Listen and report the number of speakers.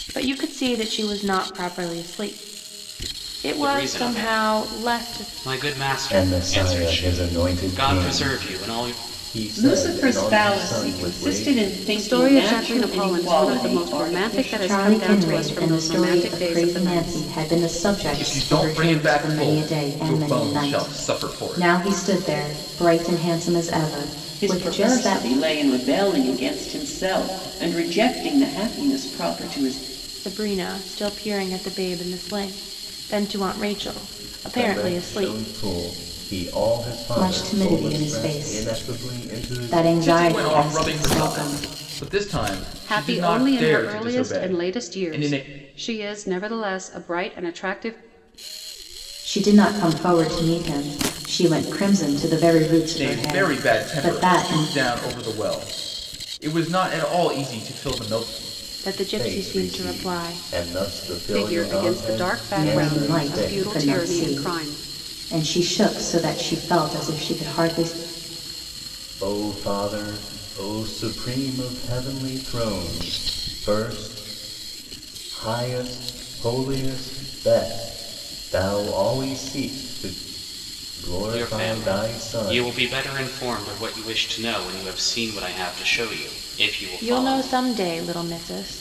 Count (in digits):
7